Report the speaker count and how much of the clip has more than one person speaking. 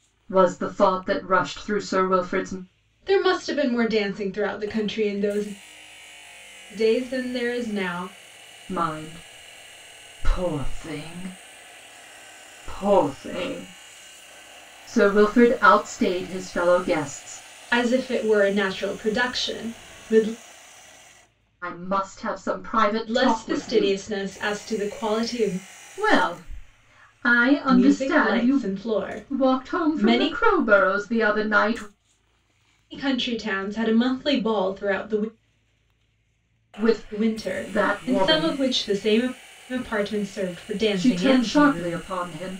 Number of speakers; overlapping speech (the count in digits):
2, about 13%